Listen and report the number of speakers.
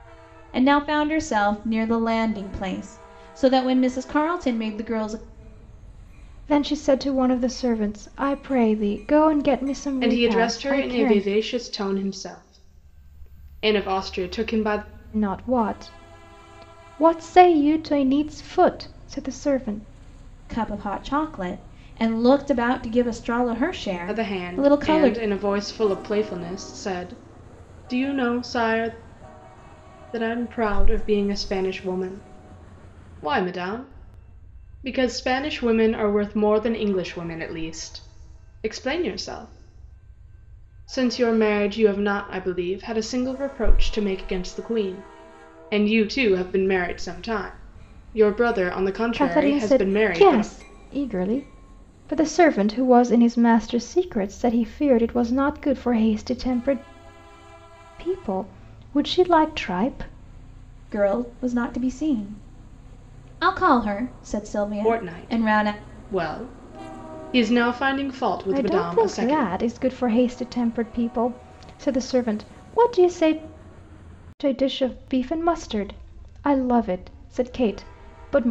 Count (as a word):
three